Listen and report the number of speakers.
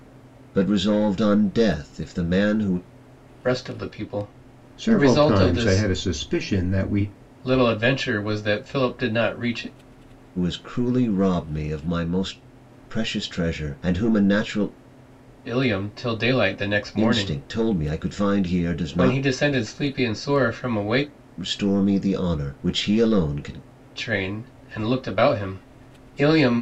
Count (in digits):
3